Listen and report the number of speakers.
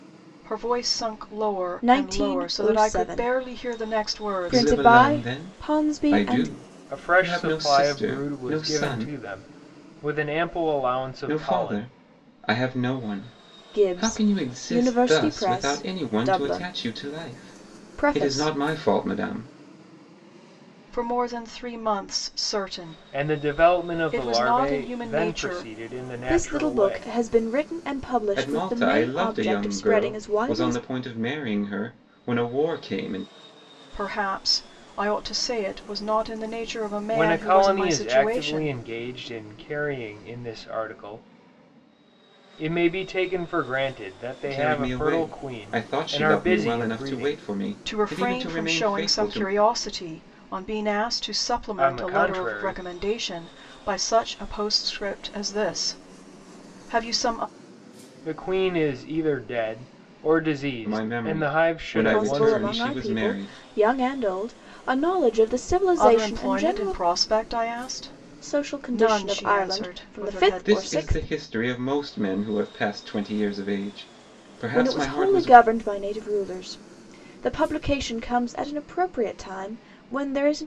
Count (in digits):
4